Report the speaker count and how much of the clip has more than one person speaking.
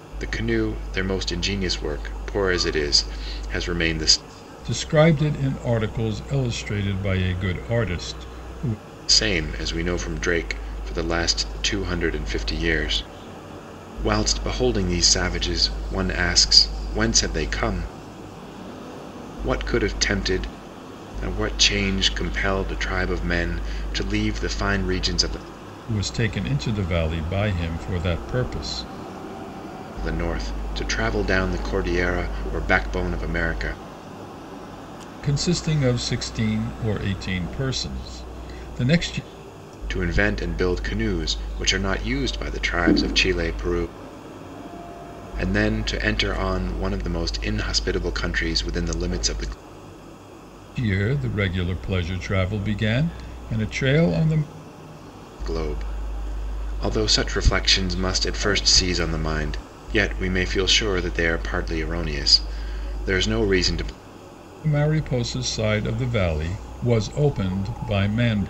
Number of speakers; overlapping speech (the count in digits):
2, no overlap